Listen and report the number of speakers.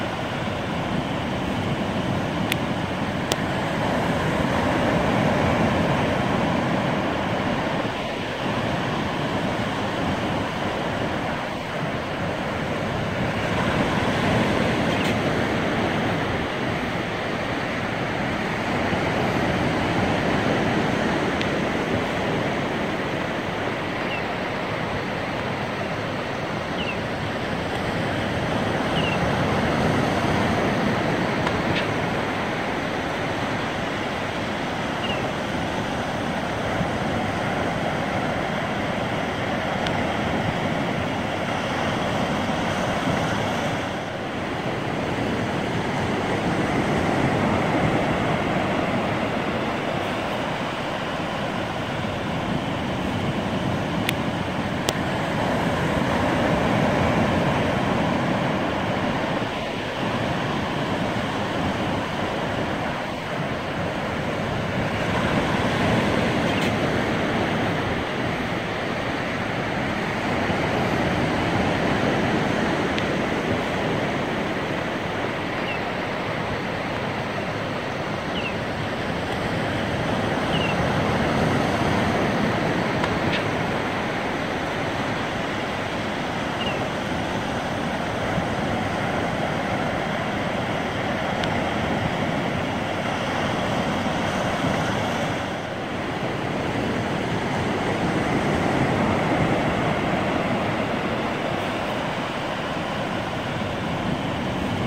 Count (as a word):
zero